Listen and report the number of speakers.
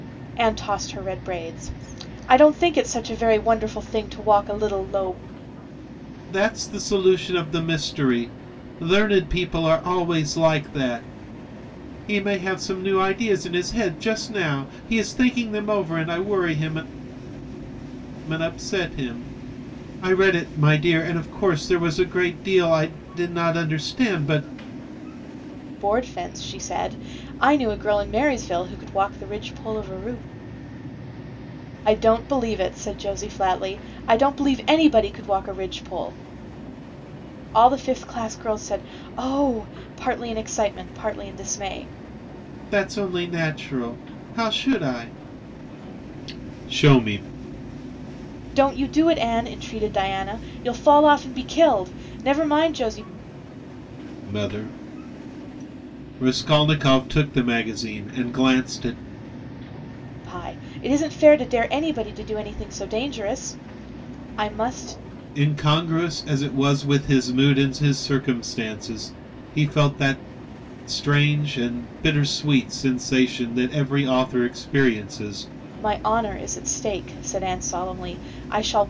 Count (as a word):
two